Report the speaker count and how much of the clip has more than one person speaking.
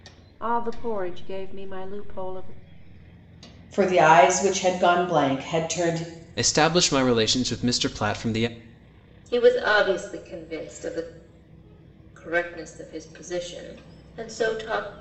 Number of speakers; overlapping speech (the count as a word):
four, no overlap